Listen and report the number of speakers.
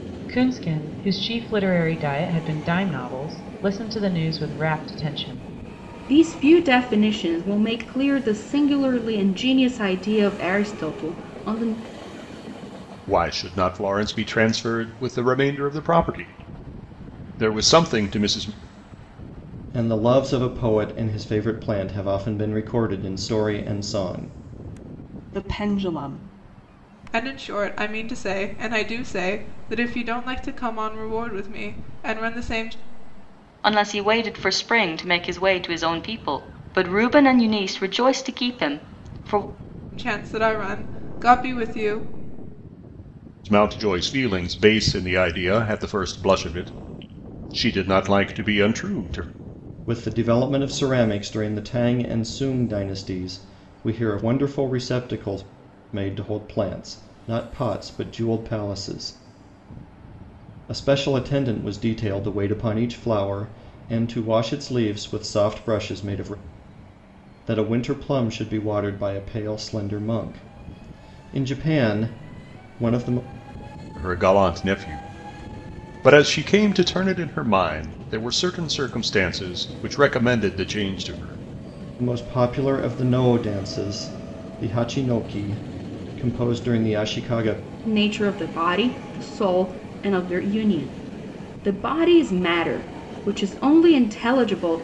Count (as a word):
seven